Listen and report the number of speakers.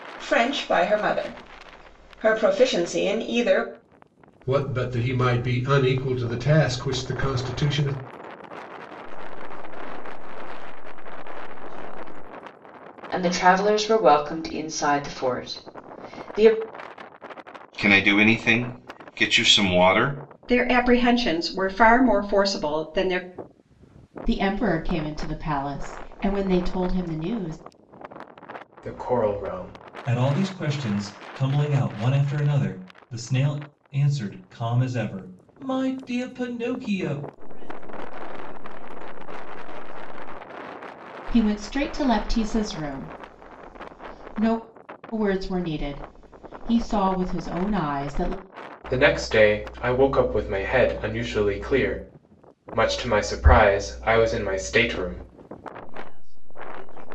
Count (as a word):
nine